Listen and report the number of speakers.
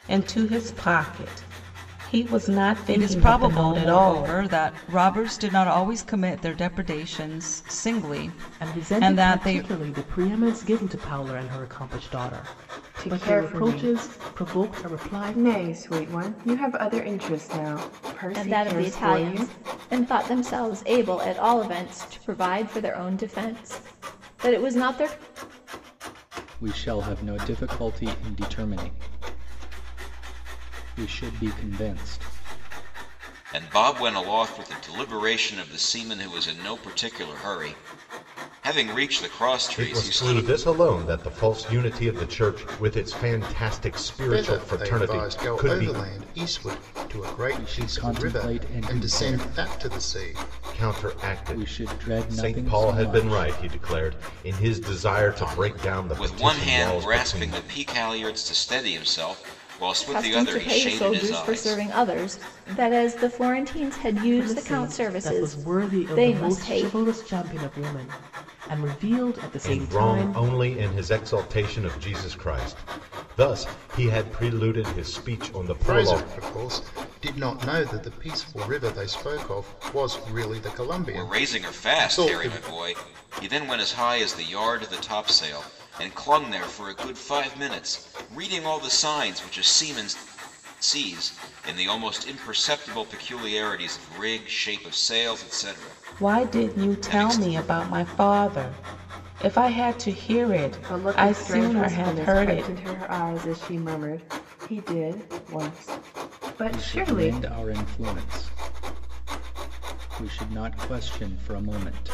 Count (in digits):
9